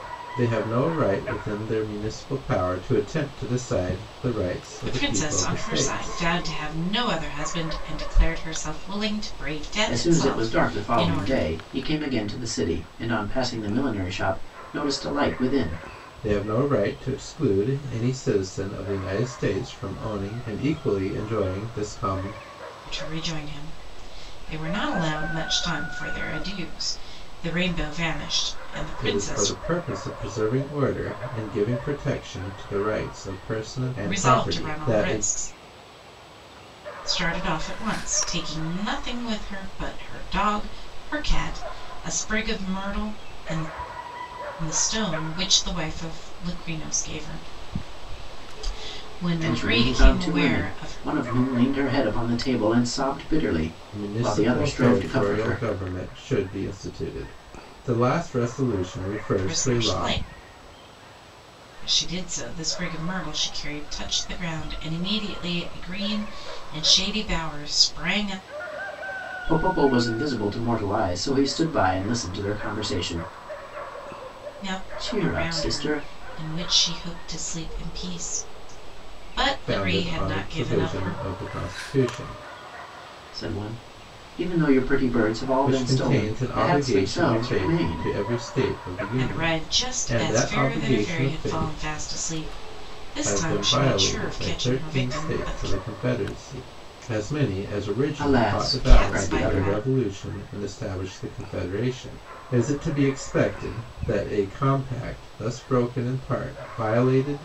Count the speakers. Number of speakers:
three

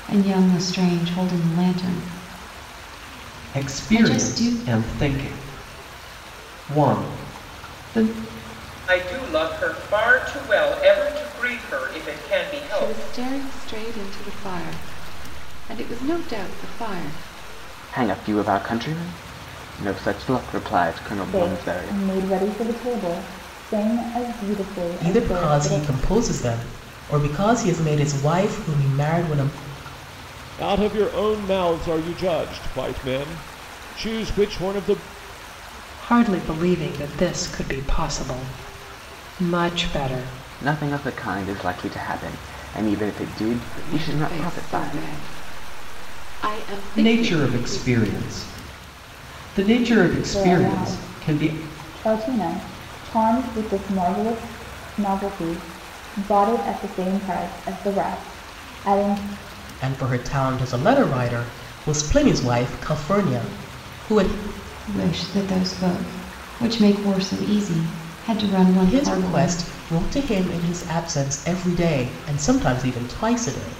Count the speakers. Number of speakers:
nine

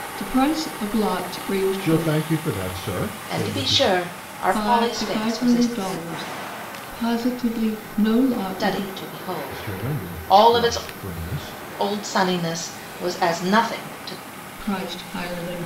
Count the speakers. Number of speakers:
three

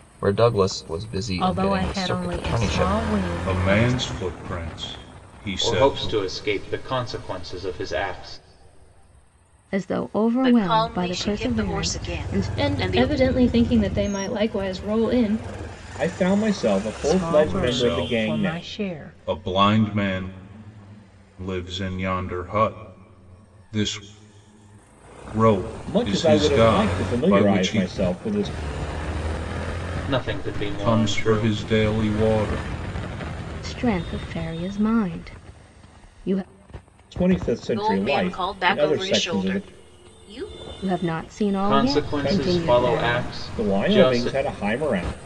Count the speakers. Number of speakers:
eight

